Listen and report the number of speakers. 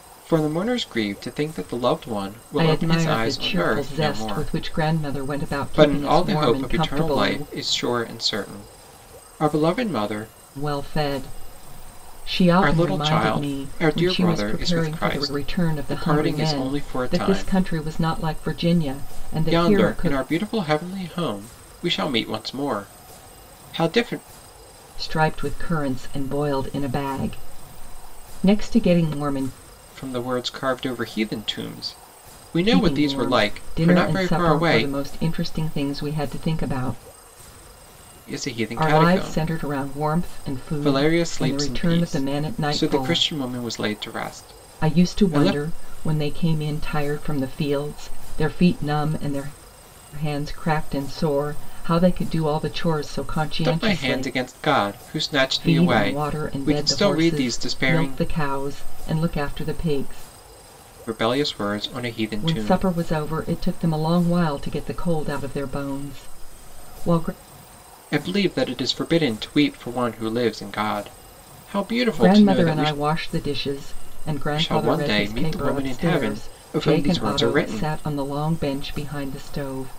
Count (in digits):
2